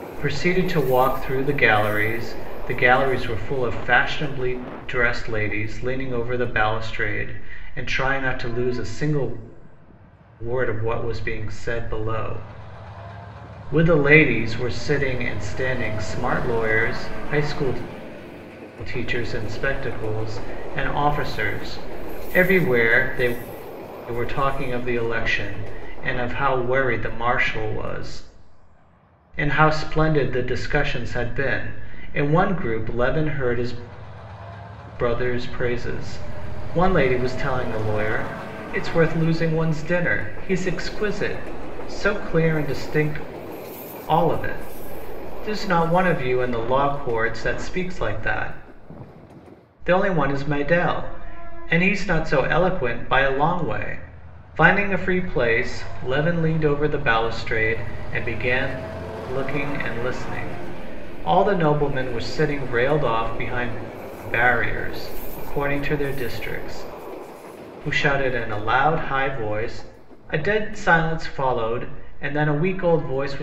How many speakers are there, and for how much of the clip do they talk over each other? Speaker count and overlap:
1, no overlap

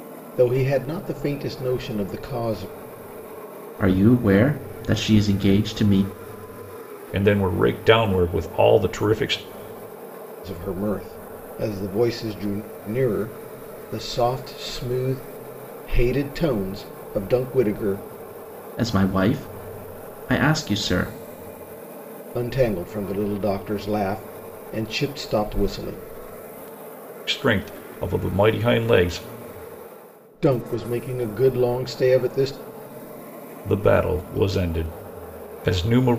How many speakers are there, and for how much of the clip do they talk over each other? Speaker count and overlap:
3, no overlap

